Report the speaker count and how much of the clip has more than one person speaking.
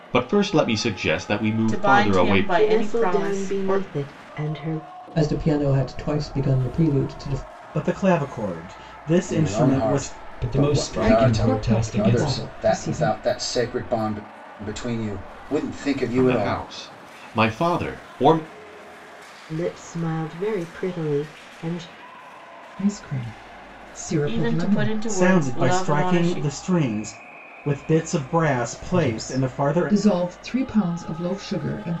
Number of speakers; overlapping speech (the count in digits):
8, about 30%